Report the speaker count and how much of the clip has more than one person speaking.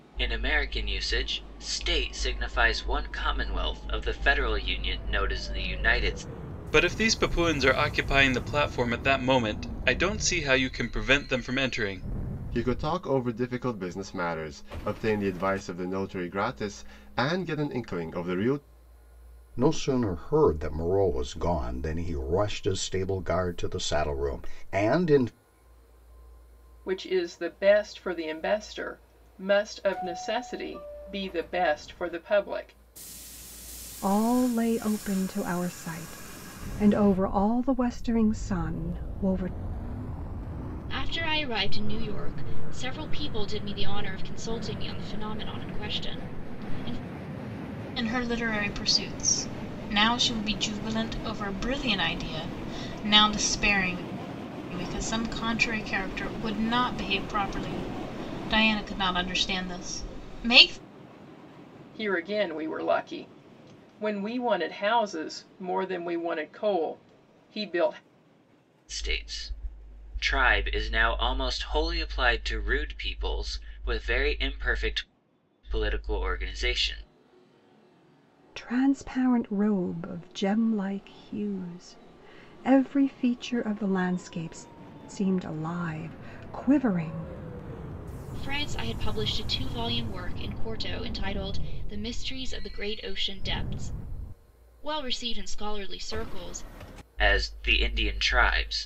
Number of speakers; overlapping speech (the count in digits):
8, no overlap